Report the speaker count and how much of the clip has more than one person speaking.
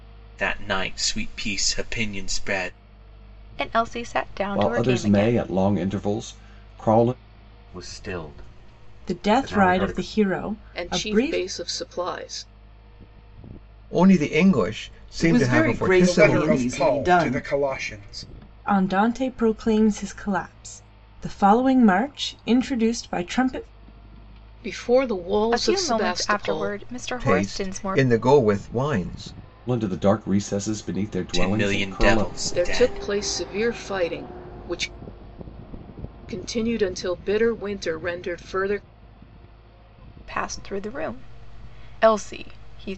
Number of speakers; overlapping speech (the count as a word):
nine, about 21%